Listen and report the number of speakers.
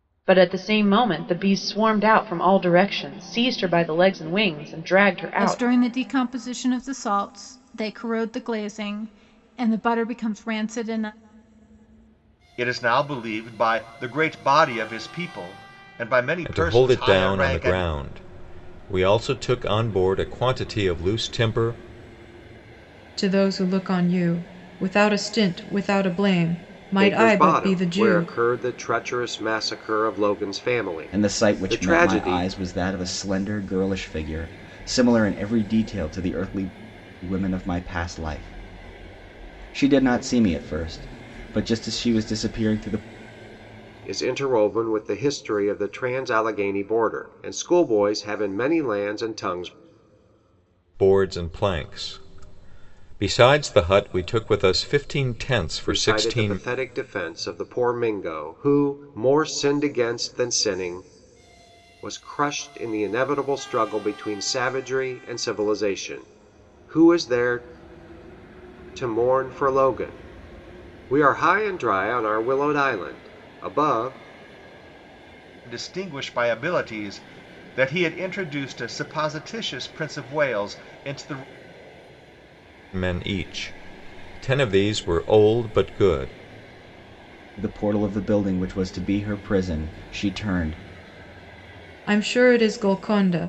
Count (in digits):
7